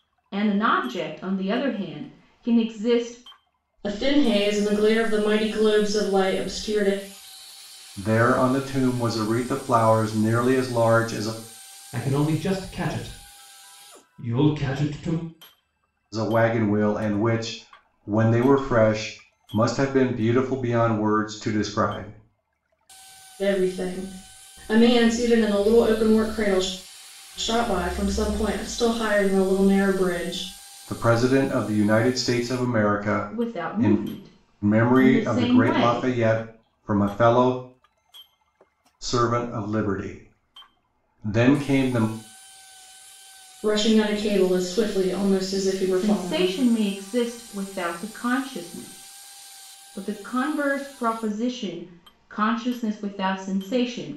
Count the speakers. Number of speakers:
4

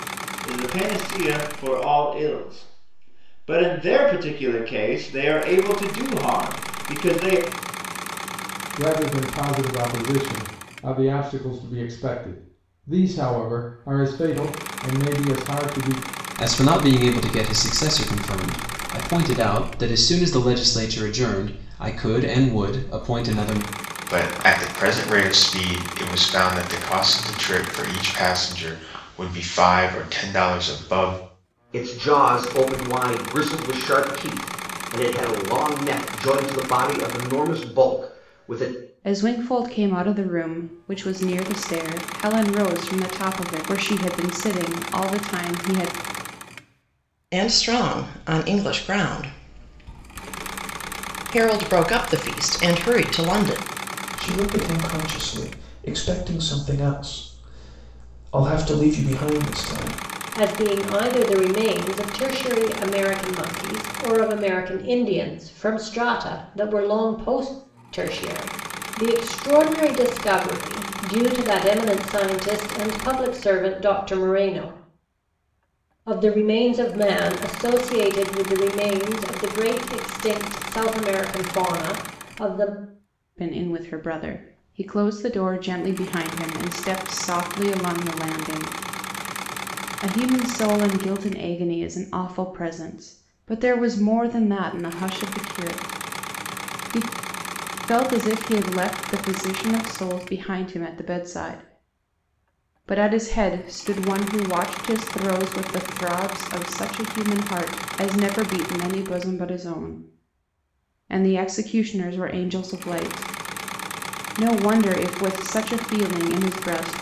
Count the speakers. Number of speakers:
9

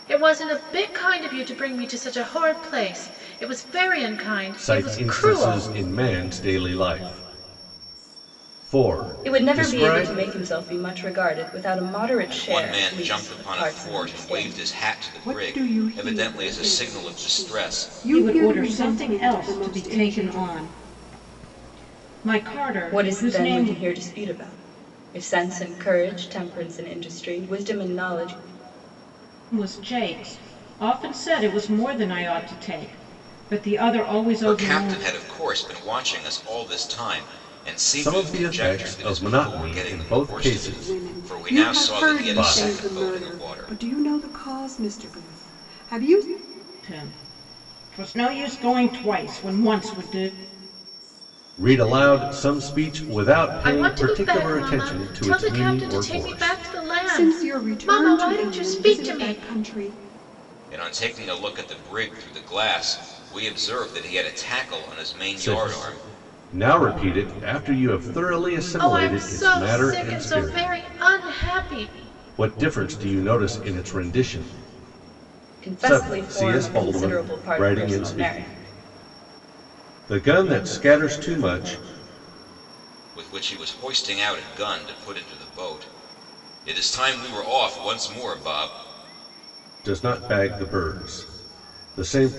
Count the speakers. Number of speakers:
6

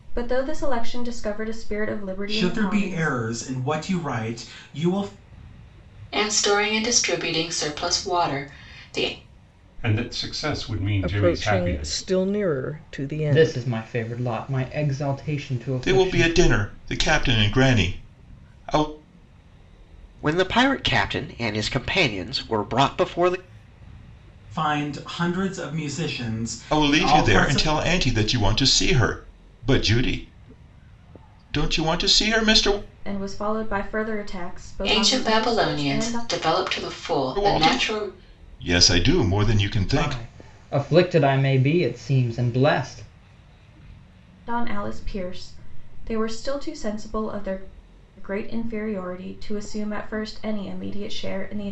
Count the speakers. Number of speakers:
8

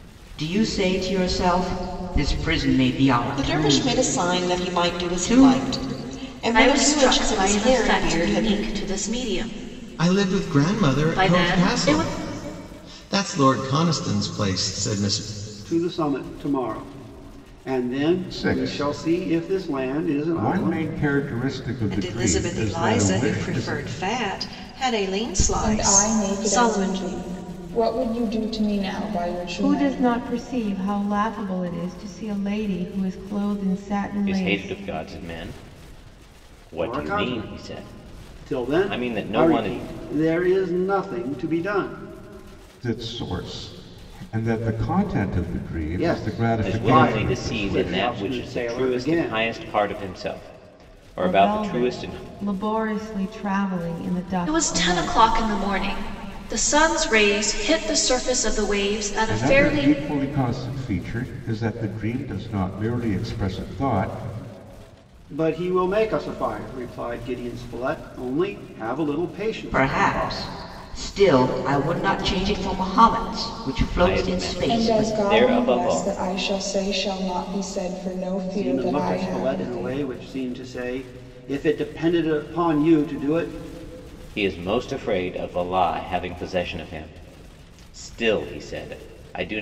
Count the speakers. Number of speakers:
10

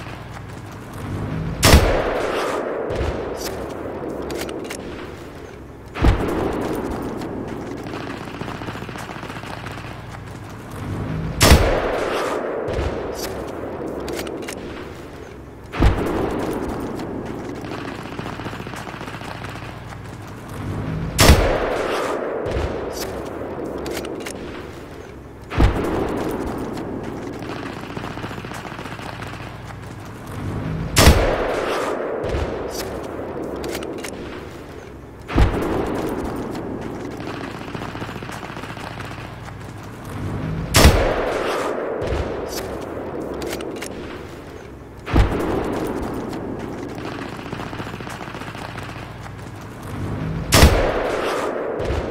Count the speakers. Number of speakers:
0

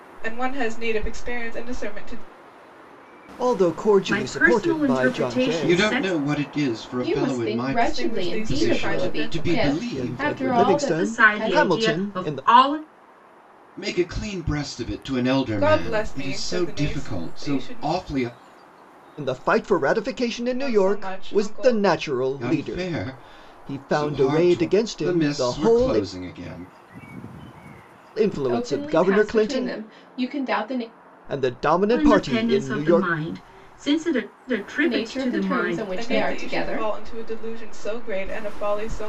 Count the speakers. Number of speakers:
5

